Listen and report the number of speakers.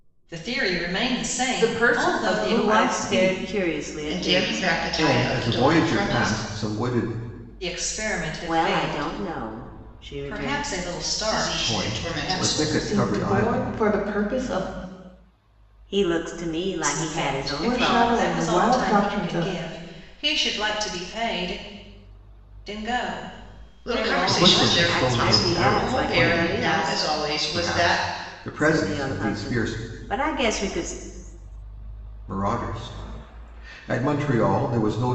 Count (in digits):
5